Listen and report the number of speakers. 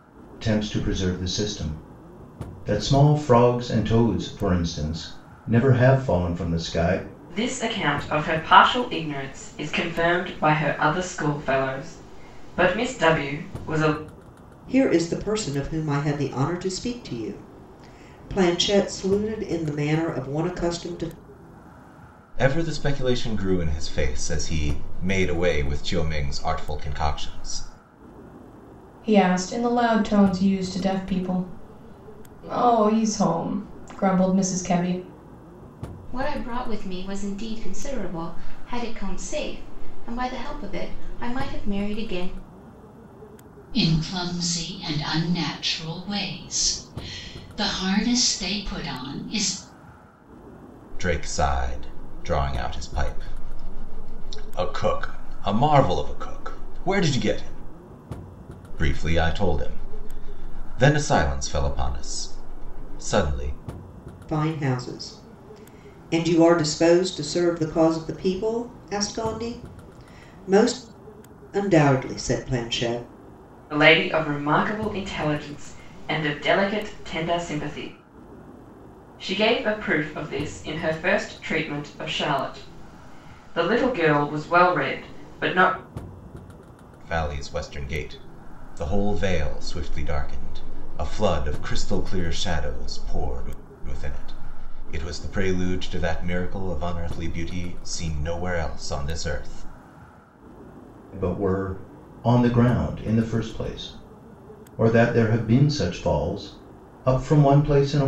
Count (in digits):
7